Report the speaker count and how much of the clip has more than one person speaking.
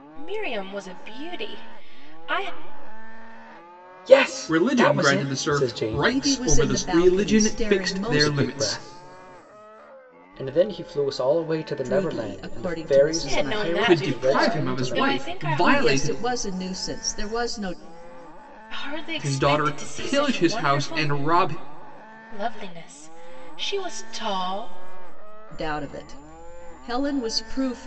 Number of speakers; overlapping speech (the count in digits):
4, about 38%